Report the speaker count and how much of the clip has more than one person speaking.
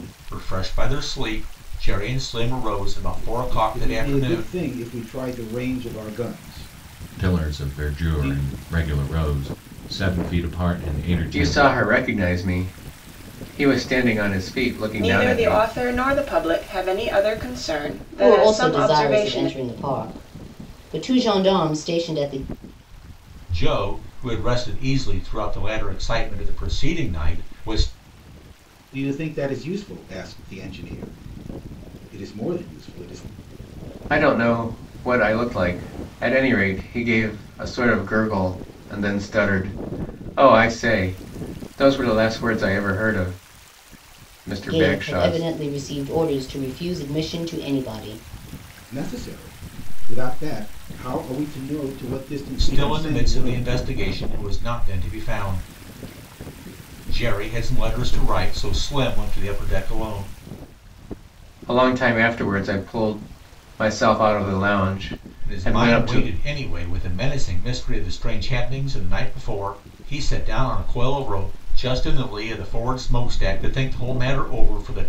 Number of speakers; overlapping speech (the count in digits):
6, about 9%